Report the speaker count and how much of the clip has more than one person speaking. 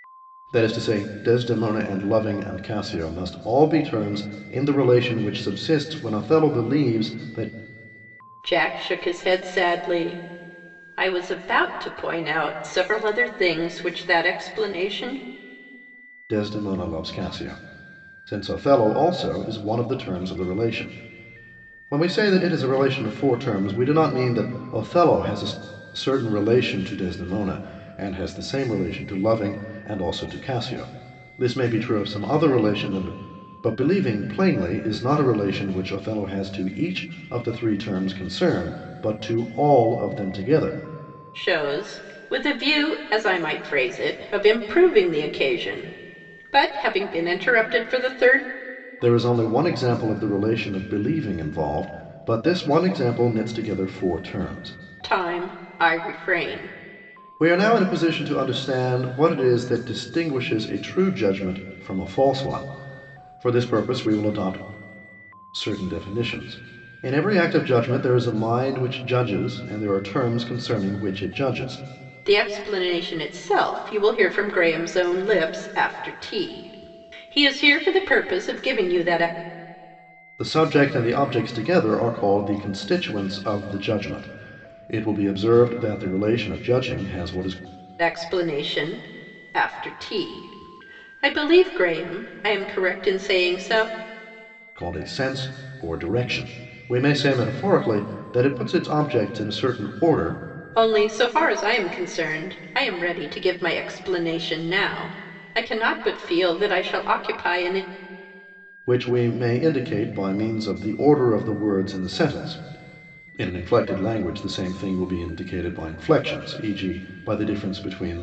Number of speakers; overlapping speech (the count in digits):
2, no overlap